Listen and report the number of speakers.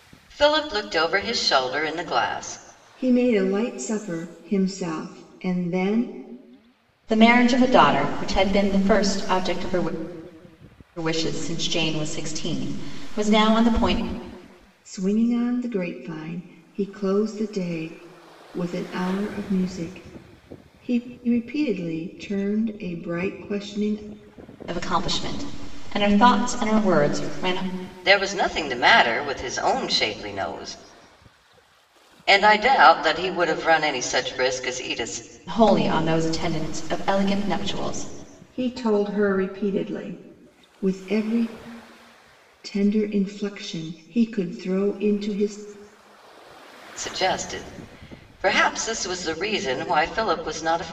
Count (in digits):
3